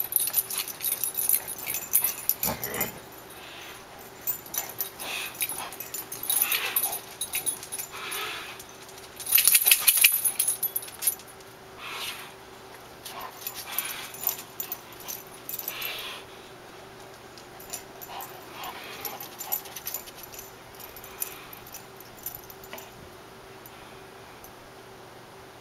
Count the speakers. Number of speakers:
0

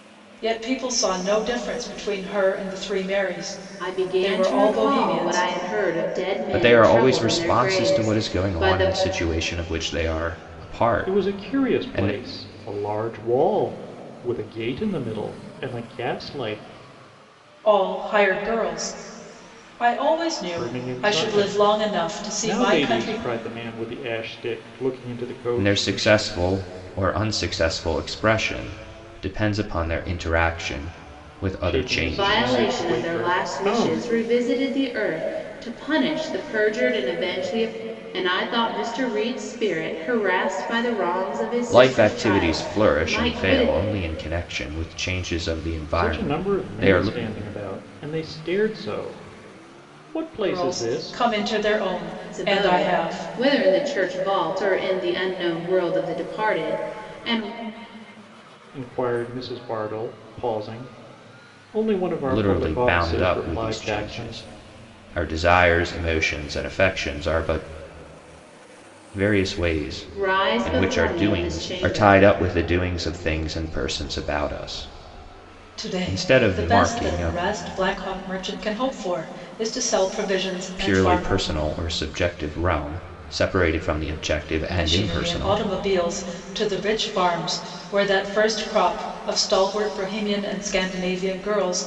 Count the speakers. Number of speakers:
4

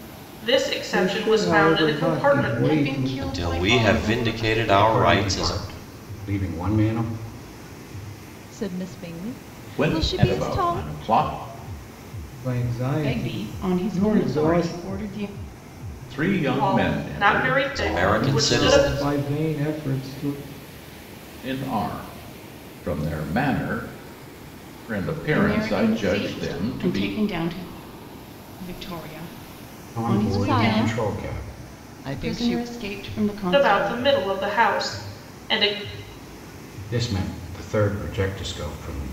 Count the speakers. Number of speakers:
7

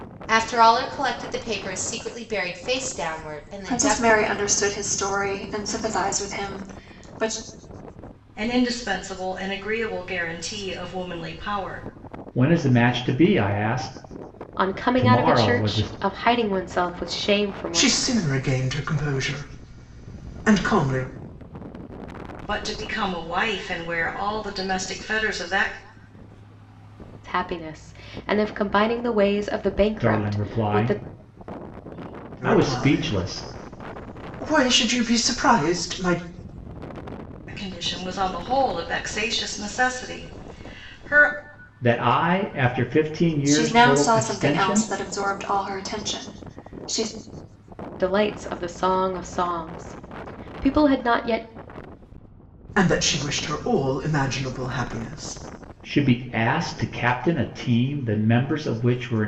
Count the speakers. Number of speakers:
6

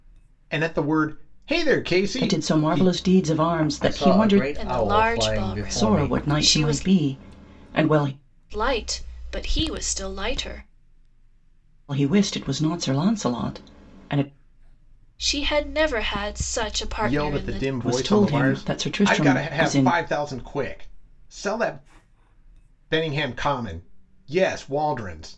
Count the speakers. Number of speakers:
4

